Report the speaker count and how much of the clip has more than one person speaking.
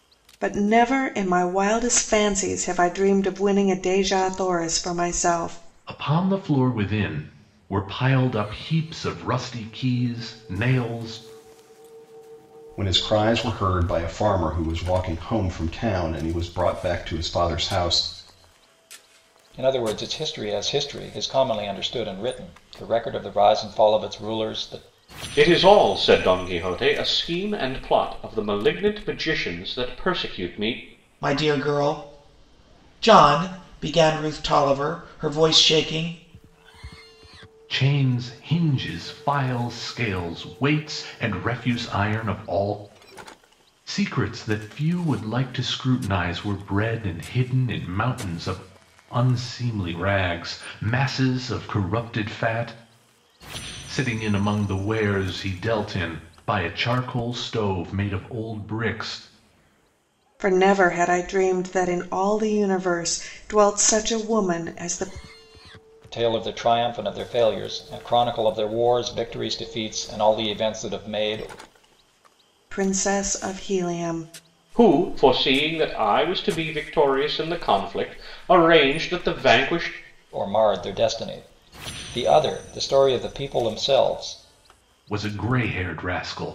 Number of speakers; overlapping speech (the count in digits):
6, no overlap